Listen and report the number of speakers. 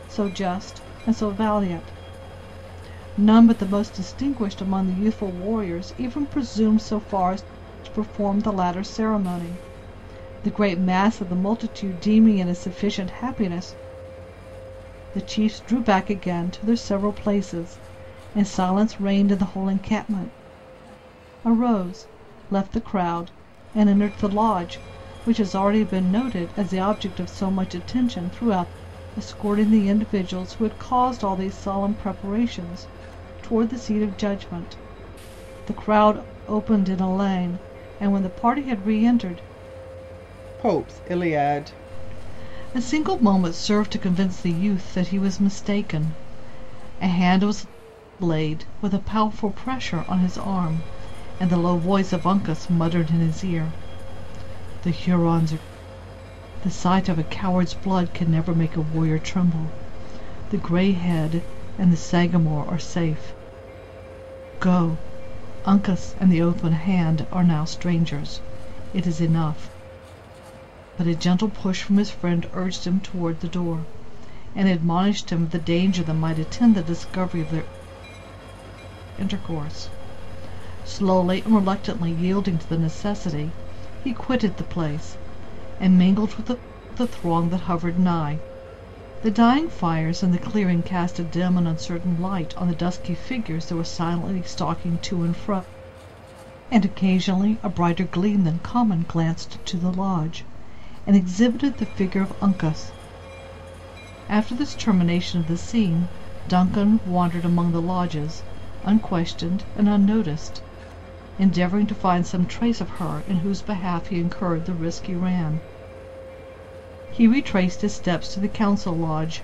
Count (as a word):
one